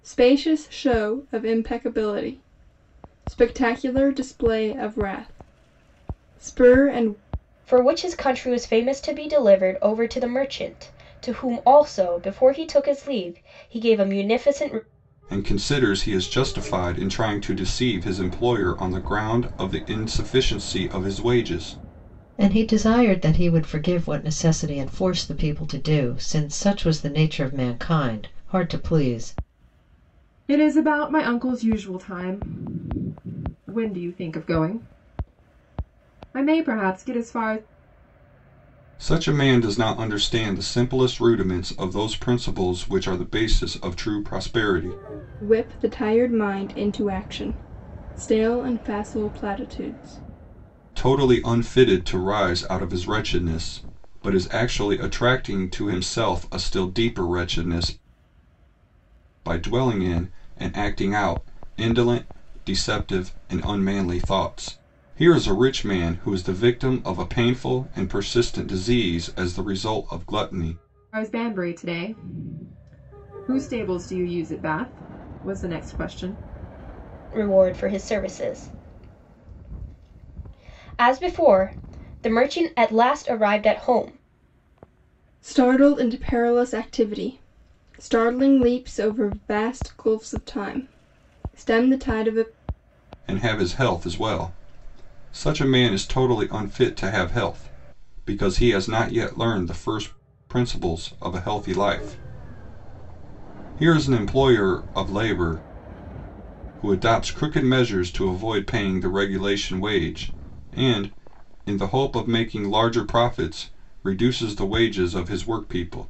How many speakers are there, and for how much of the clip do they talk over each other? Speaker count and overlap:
5, no overlap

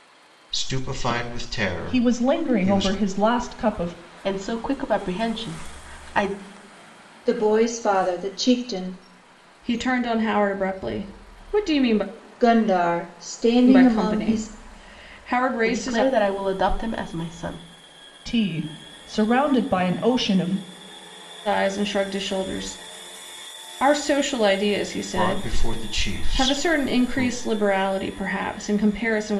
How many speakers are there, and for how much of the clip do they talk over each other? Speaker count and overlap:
5, about 13%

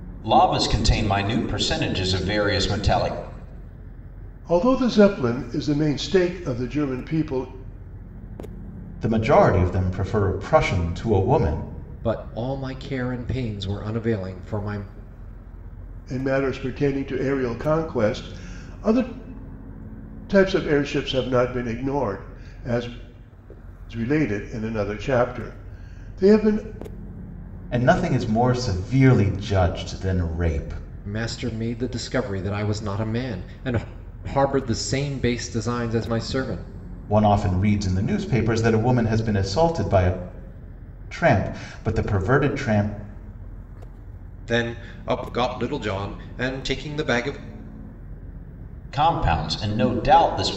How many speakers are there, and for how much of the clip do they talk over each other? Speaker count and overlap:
4, no overlap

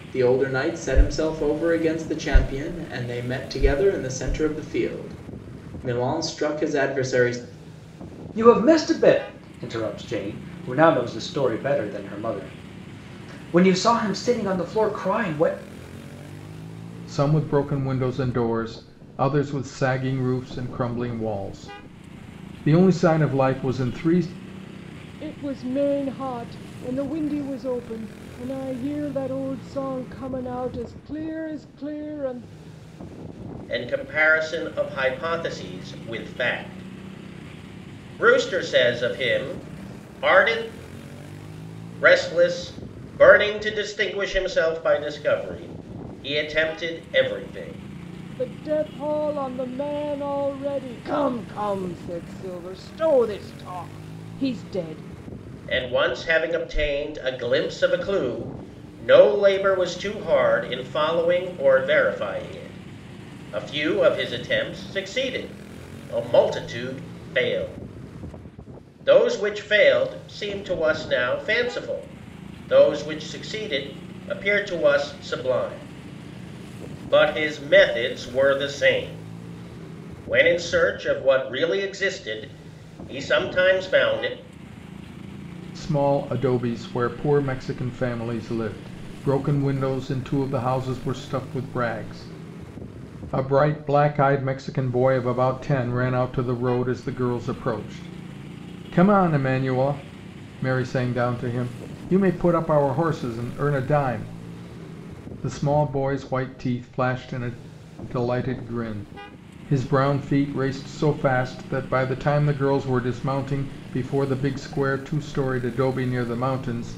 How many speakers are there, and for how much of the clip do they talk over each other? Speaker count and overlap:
5, no overlap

